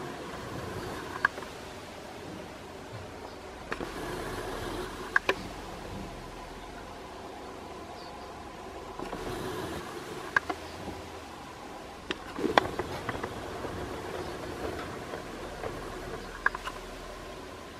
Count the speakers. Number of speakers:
0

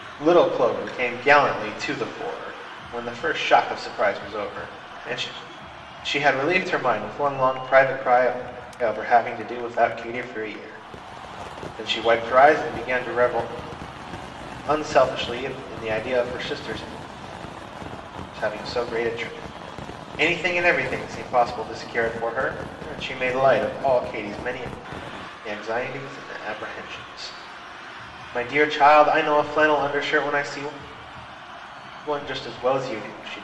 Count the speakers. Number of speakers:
1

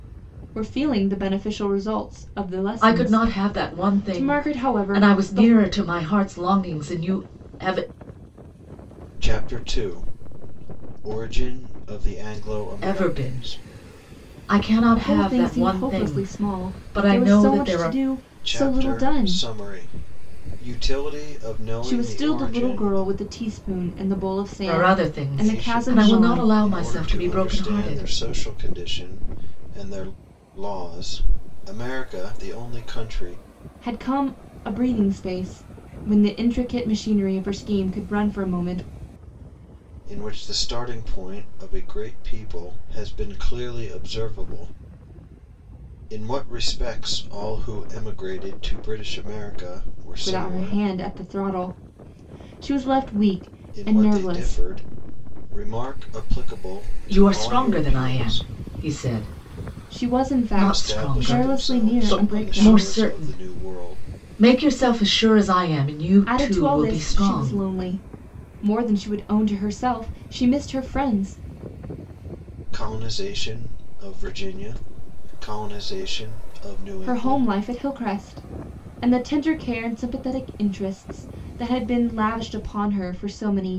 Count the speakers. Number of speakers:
3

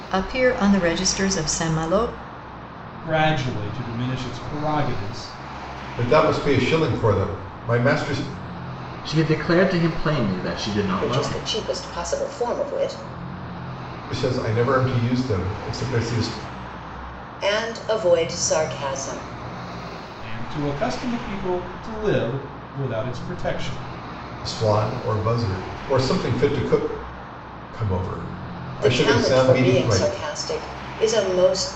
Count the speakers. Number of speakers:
5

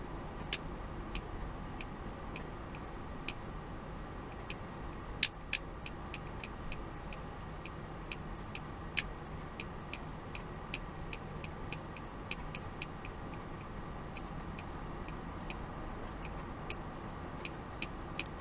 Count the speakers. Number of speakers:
0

